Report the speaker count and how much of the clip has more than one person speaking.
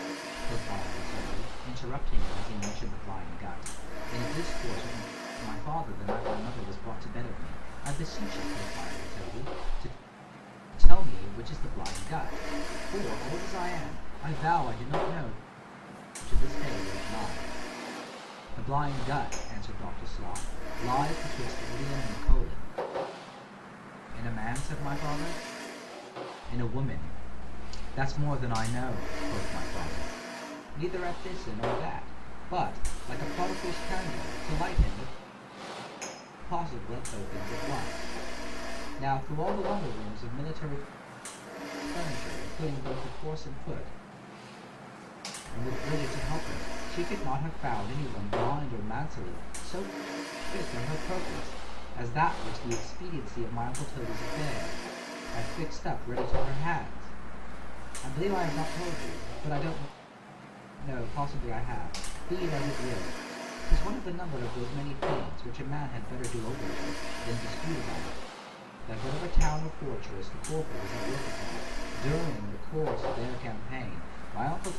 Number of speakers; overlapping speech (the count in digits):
1, no overlap